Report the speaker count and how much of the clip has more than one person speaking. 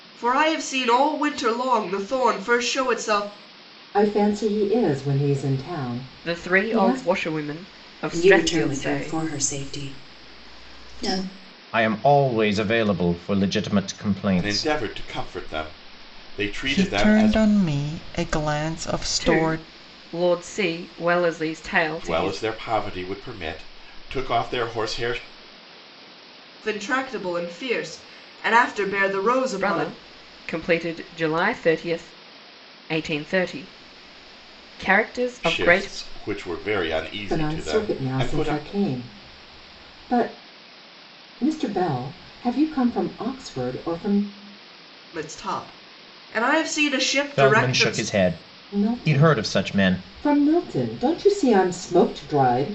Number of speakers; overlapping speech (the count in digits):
7, about 16%